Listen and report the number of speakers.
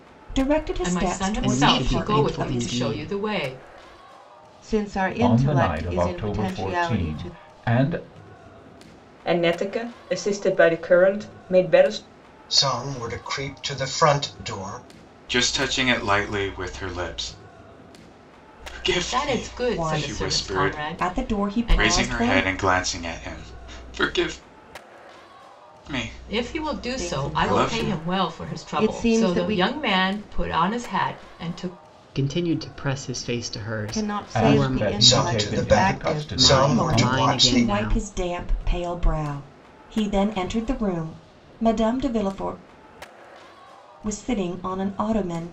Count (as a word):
eight